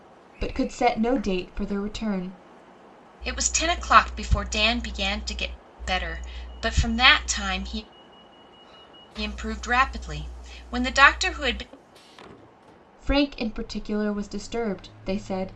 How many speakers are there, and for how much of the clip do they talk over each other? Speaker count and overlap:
two, no overlap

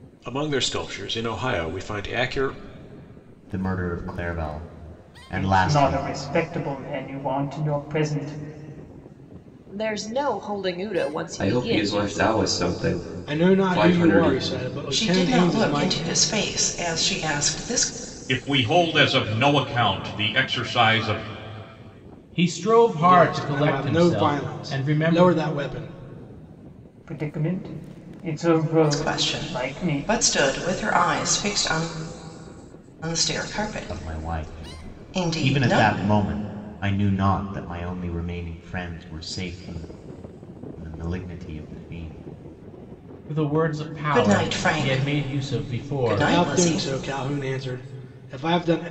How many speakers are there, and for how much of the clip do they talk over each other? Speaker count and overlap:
nine, about 25%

